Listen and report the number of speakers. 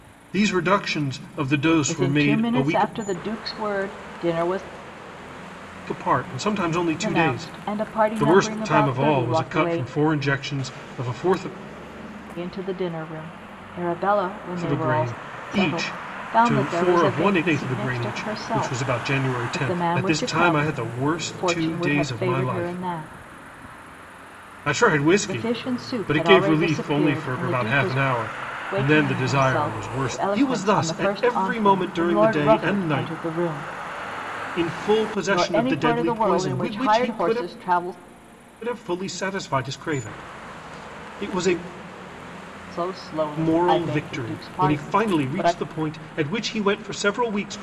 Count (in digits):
2